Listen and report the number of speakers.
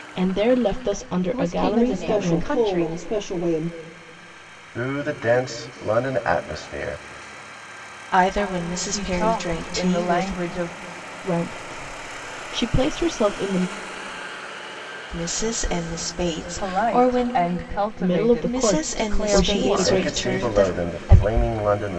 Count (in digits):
6